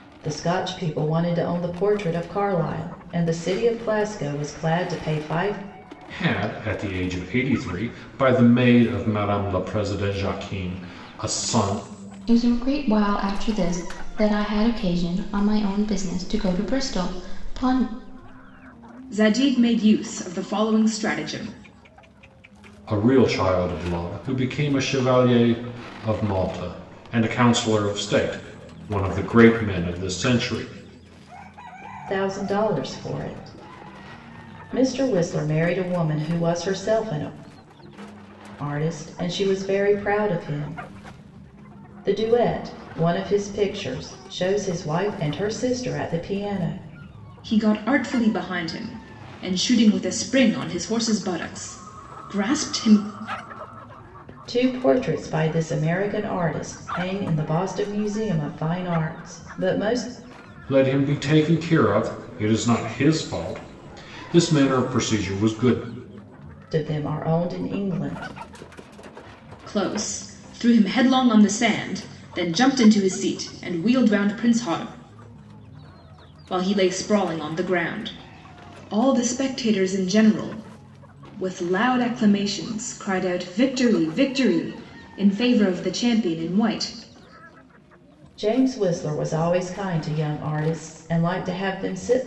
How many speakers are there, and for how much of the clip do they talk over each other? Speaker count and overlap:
4, no overlap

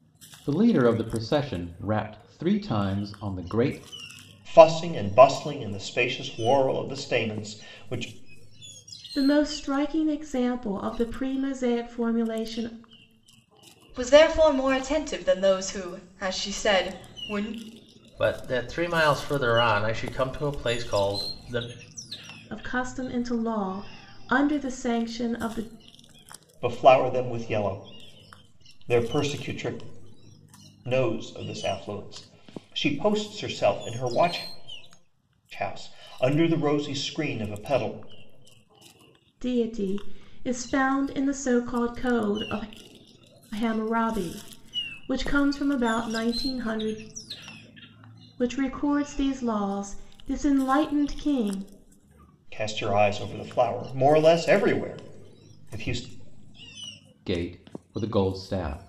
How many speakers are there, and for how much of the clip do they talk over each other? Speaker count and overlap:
5, no overlap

